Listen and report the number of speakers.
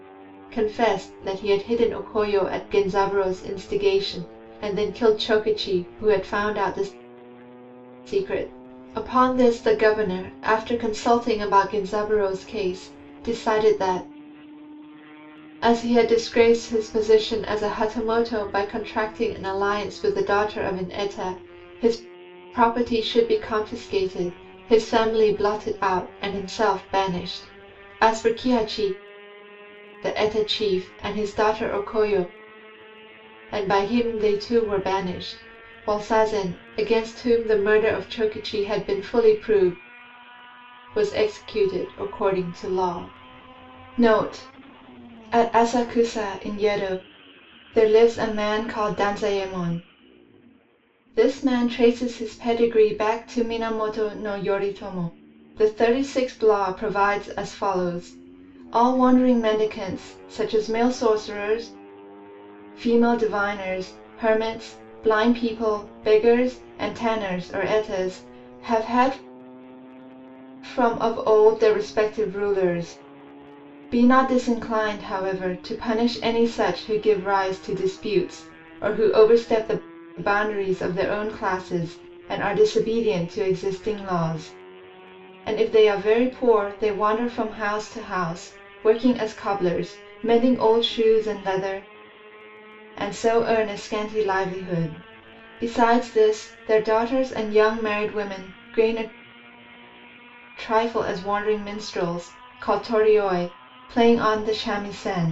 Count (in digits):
1